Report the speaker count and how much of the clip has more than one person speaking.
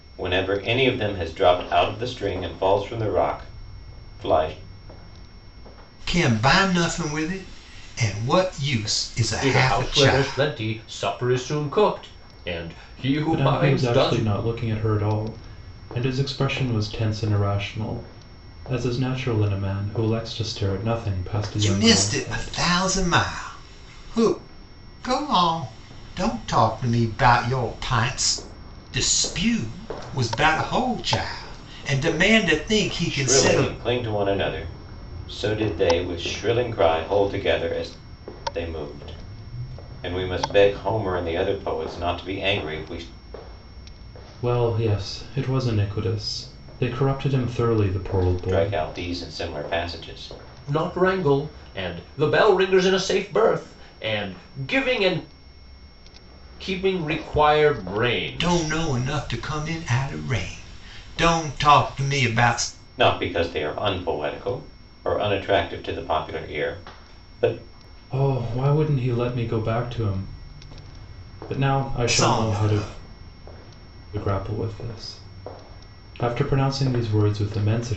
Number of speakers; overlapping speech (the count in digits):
4, about 7%